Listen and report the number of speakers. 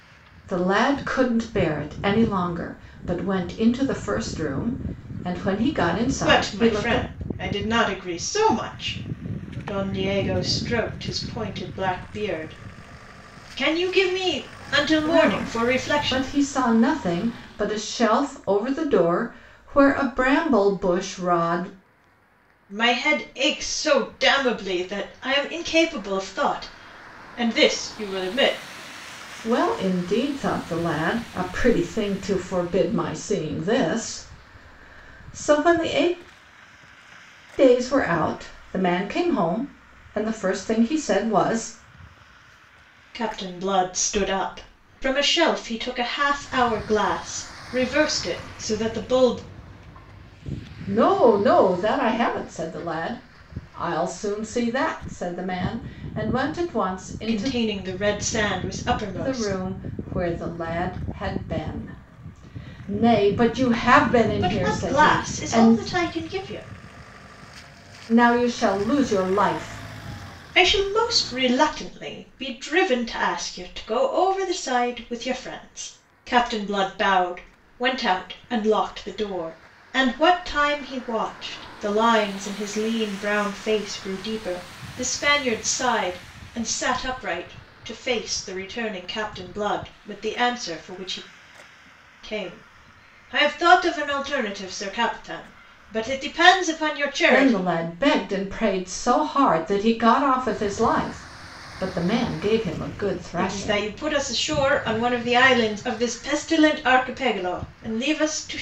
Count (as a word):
two